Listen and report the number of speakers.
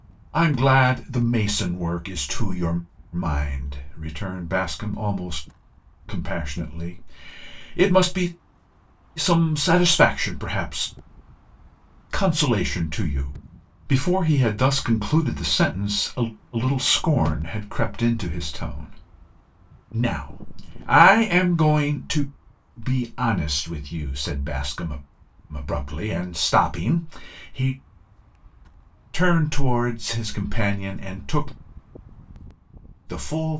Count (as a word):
one